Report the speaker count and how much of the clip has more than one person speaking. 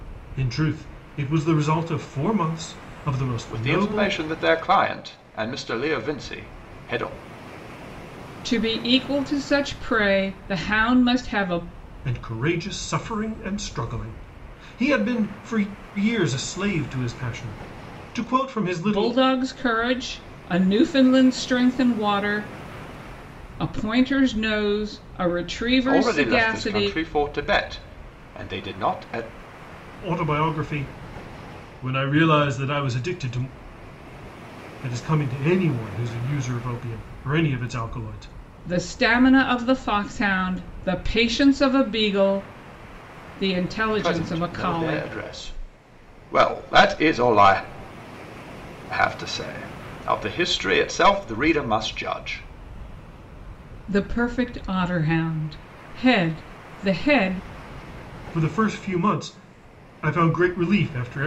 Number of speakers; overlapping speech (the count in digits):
3, about 5%